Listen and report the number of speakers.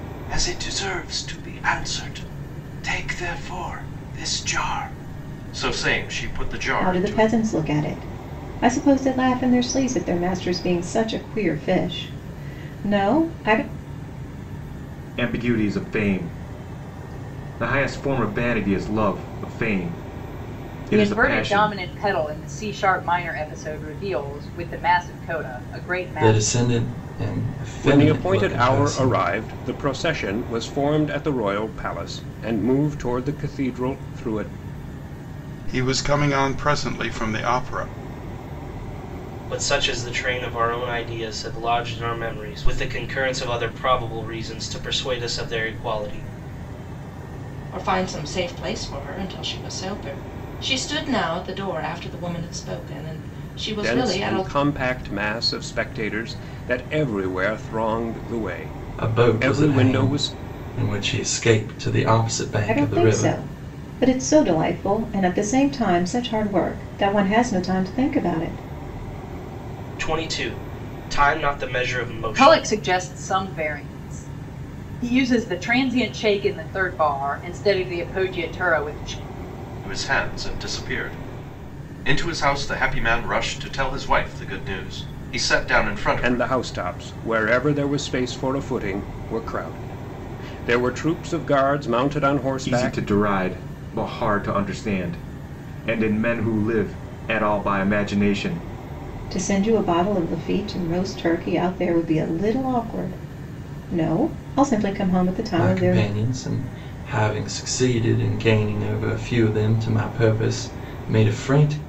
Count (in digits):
9